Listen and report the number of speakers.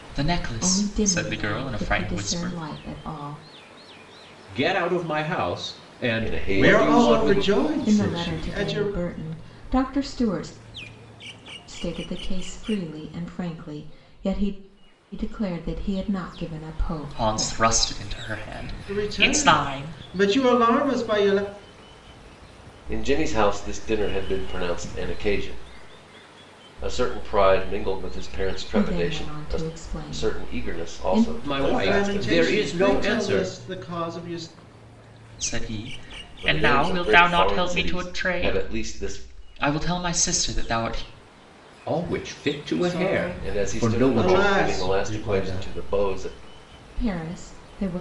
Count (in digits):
5